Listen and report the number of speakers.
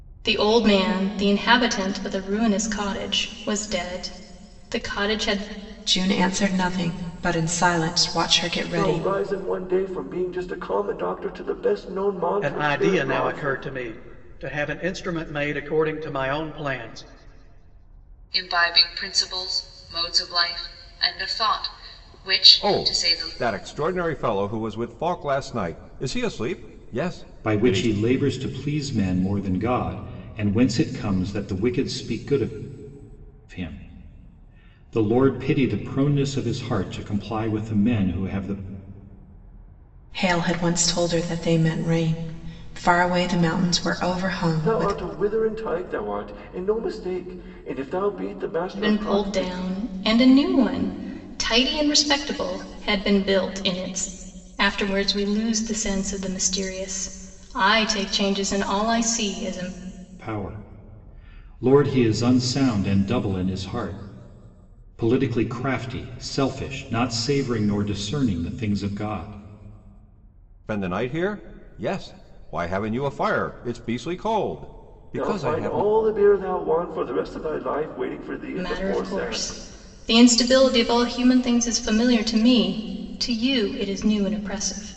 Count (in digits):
7